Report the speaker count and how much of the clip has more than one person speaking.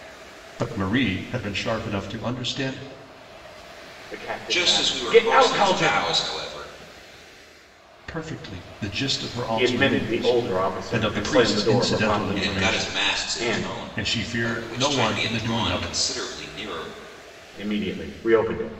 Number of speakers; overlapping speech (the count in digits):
3, about 40%